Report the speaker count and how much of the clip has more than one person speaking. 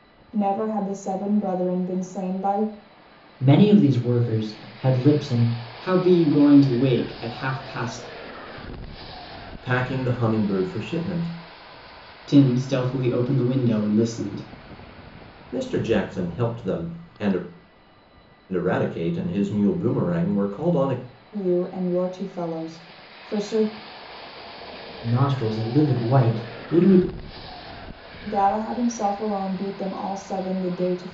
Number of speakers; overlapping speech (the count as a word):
four, no overlap